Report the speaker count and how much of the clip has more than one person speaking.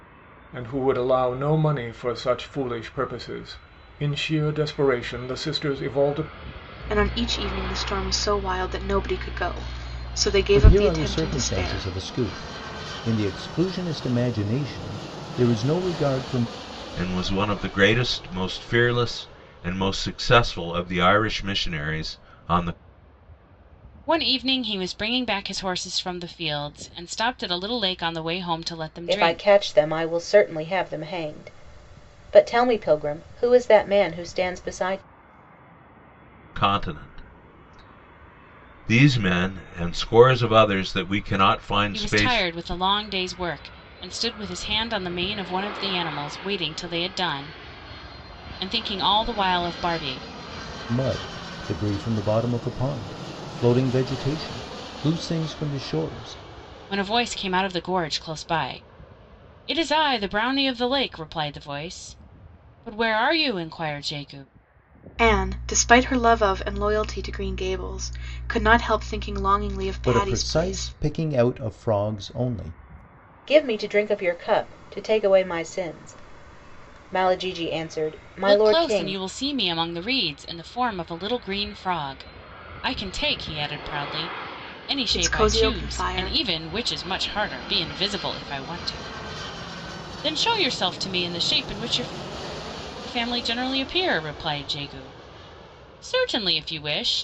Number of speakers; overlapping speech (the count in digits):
6, about 6%